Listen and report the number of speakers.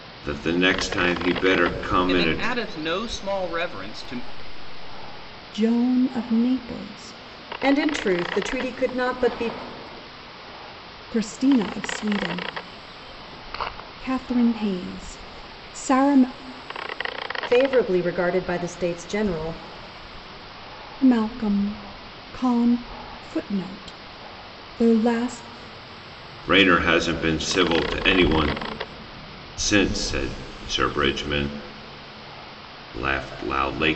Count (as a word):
four